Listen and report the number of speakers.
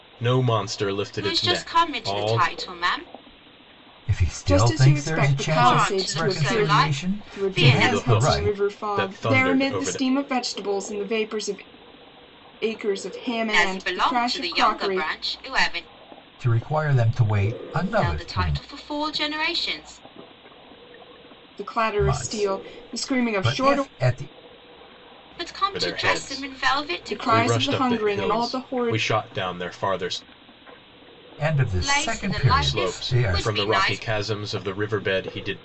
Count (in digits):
4